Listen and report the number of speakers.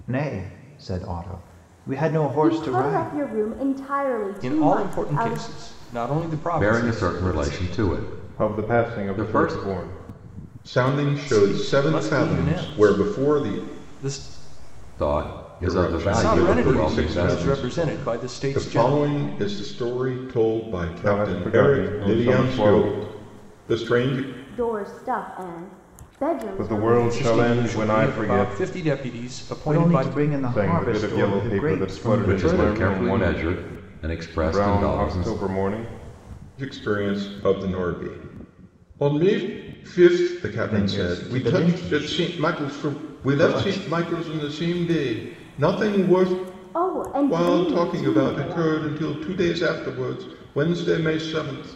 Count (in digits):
6